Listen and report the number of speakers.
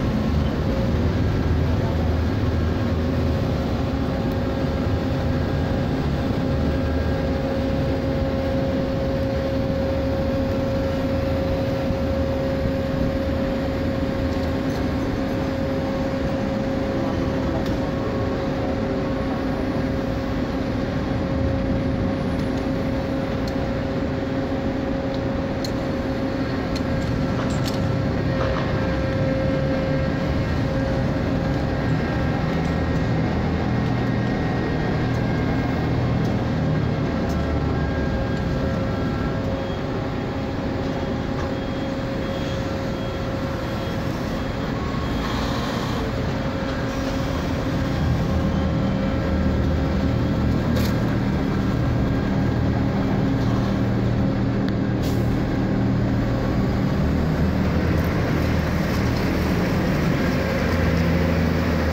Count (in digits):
0